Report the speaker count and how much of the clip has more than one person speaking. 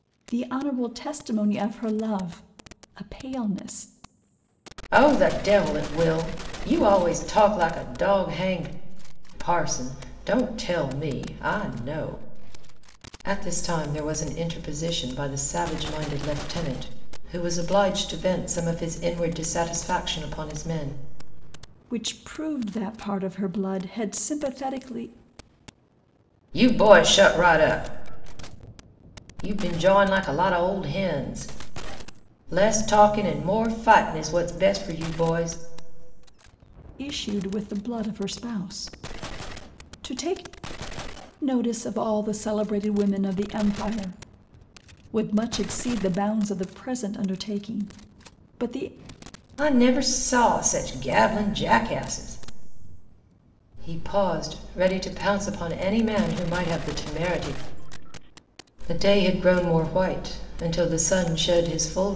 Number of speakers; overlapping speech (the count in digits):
2, no overlap